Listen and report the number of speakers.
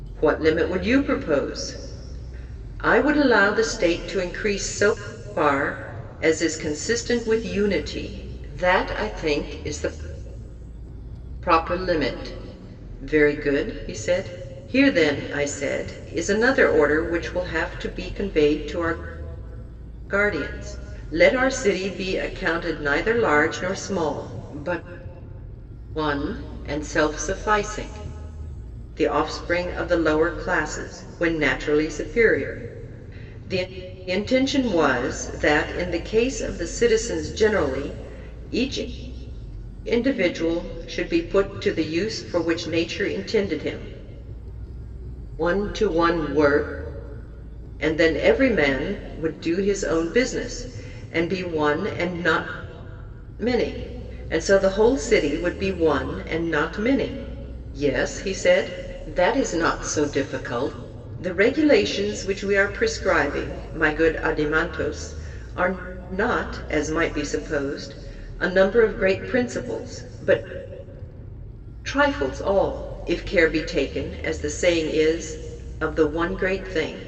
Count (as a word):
one